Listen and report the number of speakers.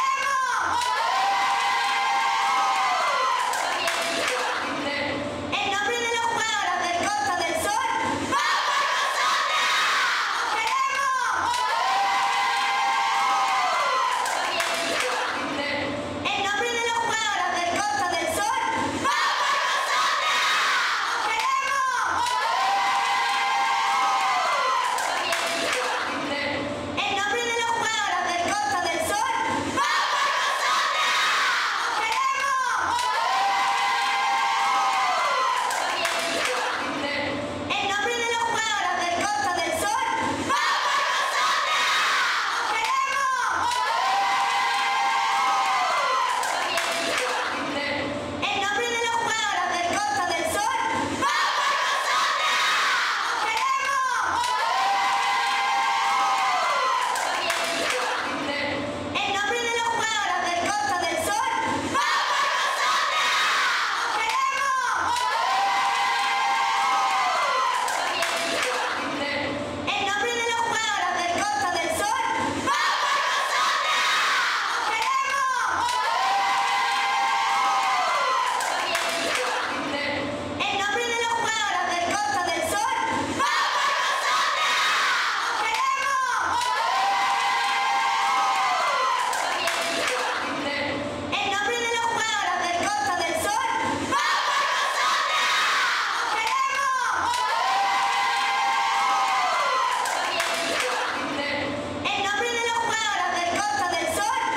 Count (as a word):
zero